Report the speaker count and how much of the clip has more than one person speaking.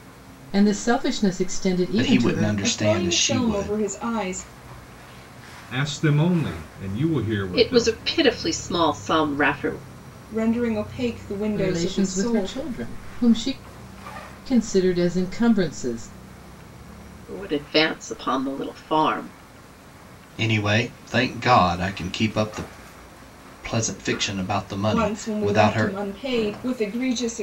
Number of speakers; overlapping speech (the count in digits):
5, about 16%